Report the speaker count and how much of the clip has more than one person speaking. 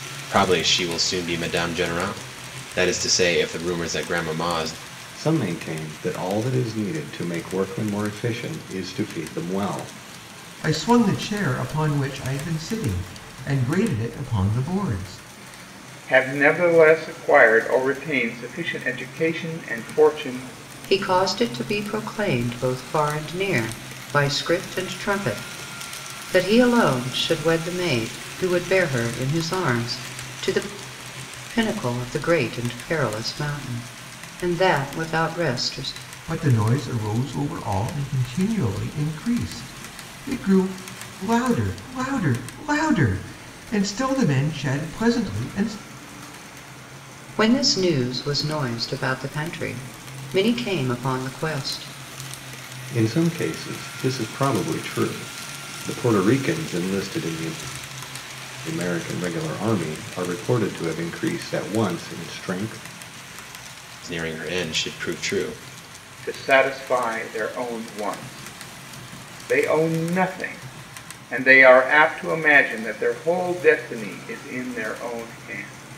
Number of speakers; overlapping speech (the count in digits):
5, no overlap